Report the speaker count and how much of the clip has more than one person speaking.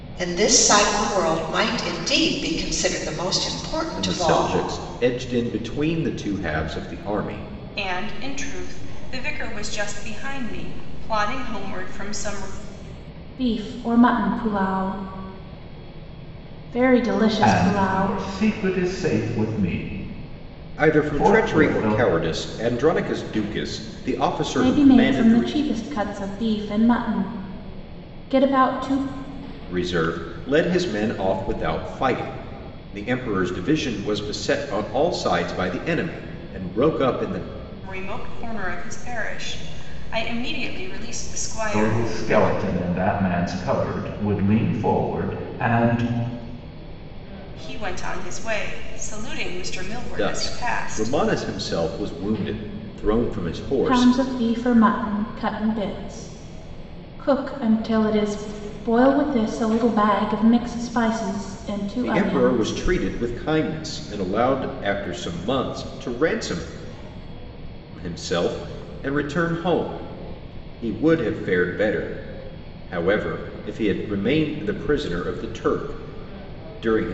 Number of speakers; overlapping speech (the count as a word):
five, about 9%